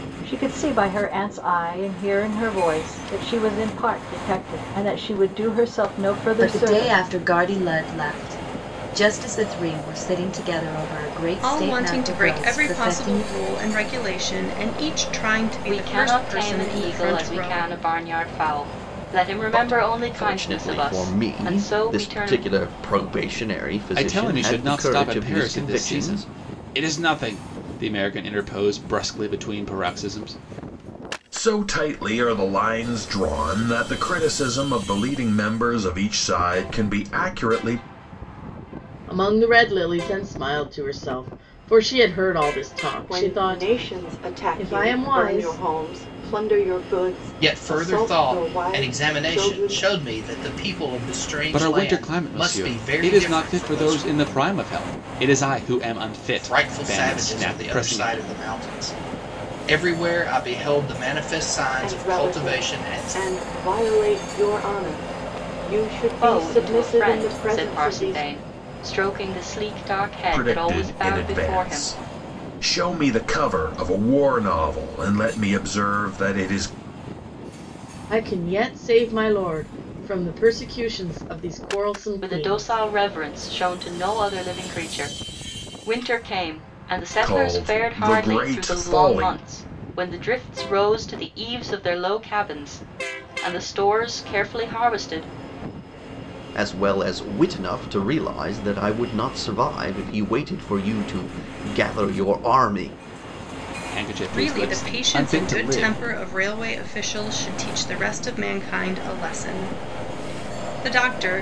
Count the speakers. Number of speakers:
ten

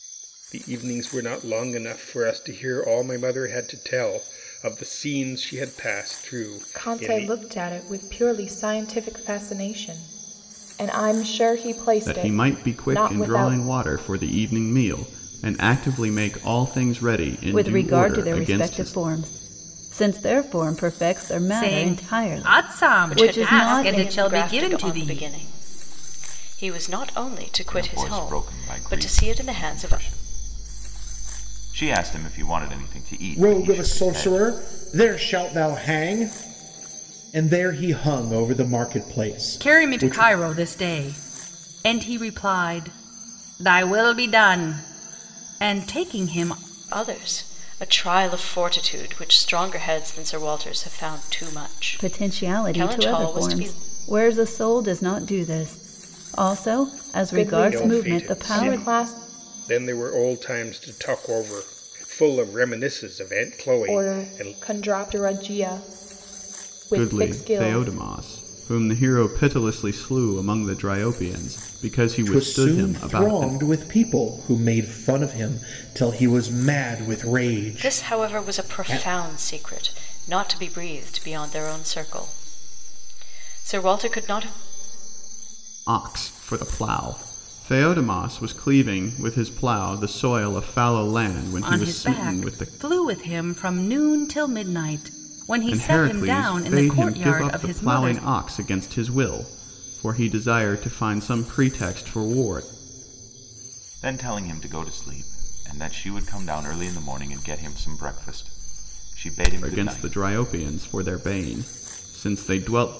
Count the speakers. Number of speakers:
eight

